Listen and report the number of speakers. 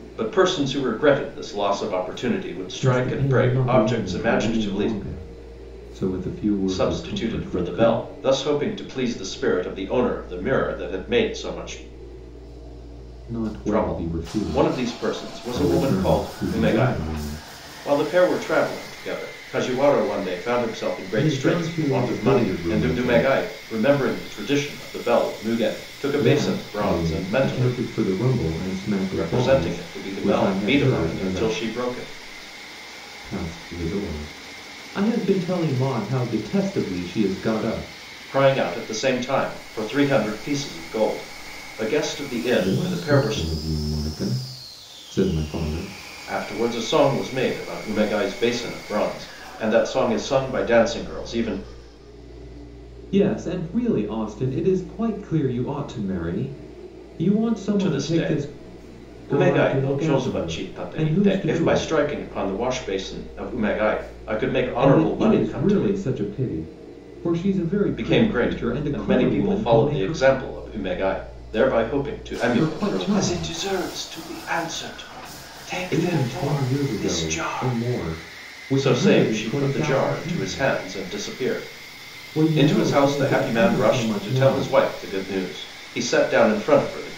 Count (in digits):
2